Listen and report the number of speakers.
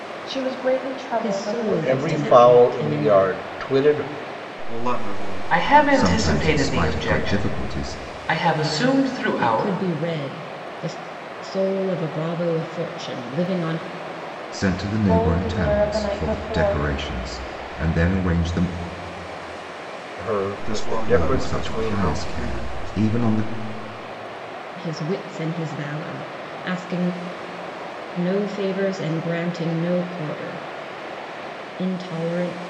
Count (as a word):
six